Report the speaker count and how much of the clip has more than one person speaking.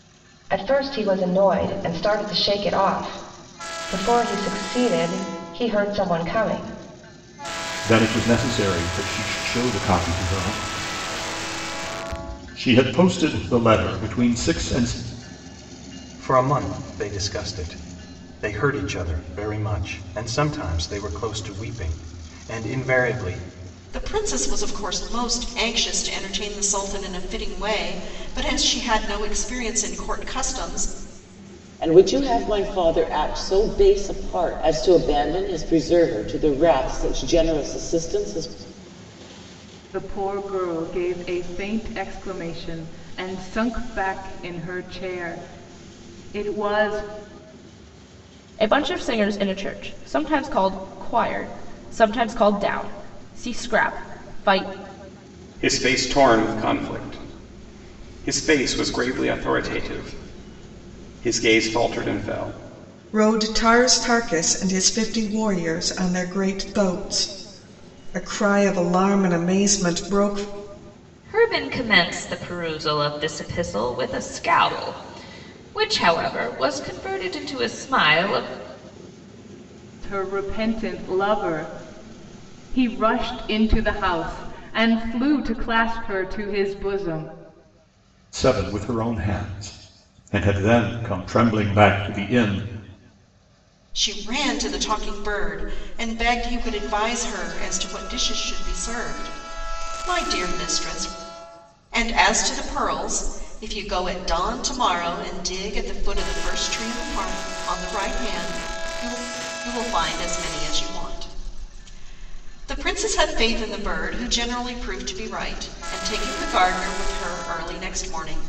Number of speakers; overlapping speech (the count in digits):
10, no overlap